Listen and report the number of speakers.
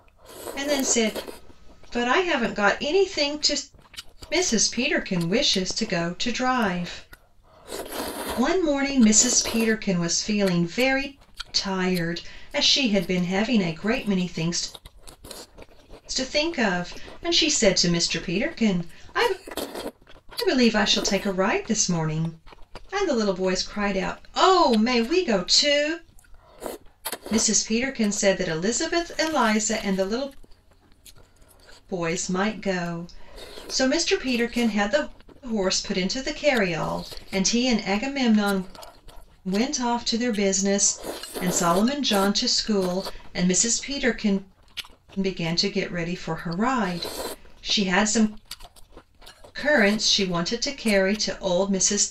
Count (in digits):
1